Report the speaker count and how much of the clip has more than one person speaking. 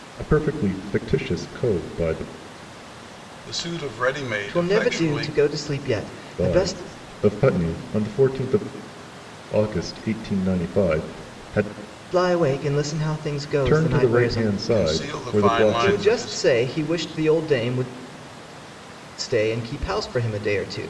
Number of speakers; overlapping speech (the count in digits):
3, about 19%